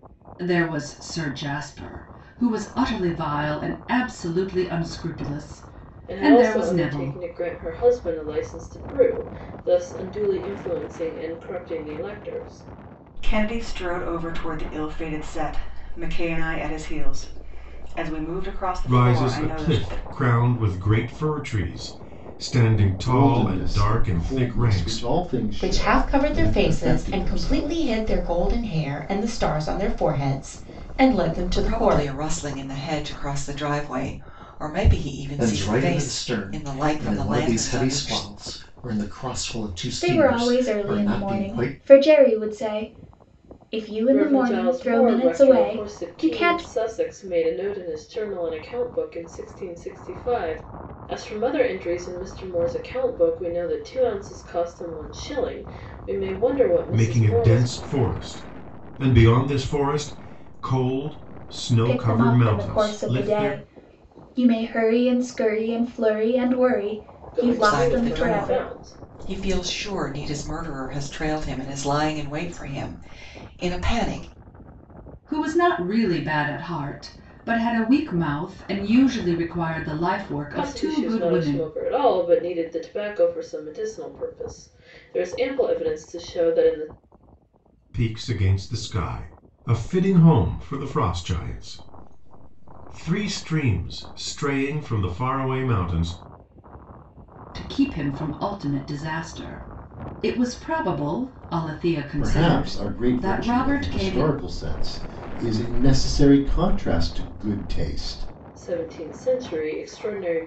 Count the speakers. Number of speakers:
nine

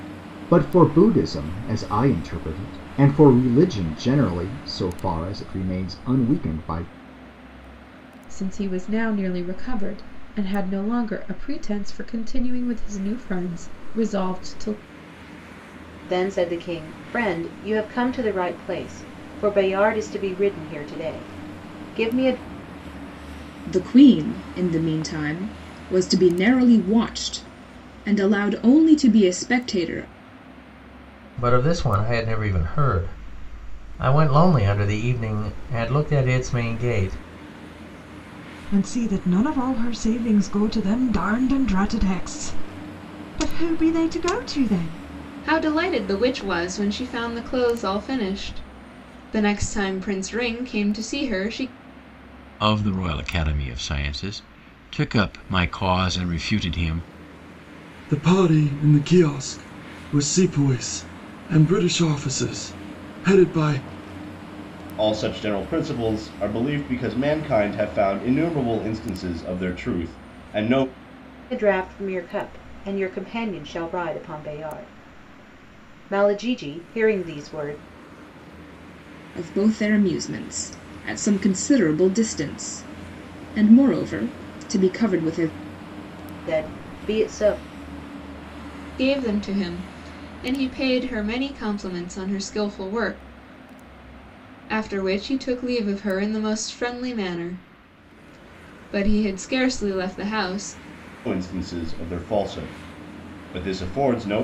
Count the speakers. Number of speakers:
ten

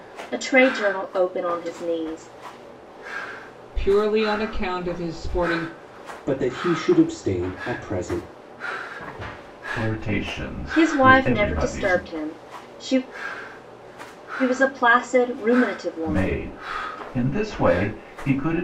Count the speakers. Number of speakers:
four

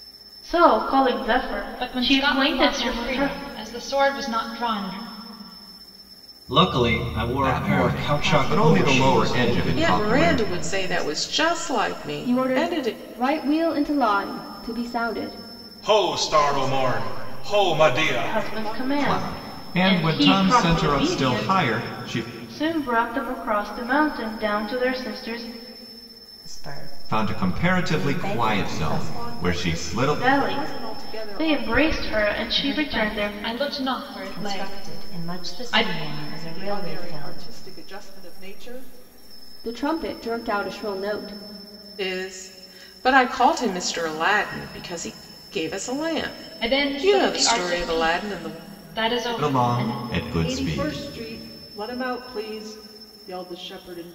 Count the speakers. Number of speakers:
nine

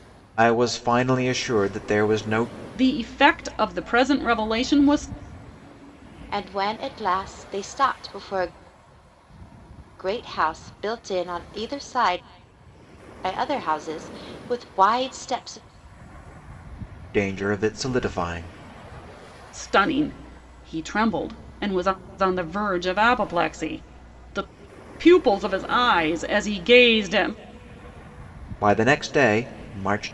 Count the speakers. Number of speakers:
three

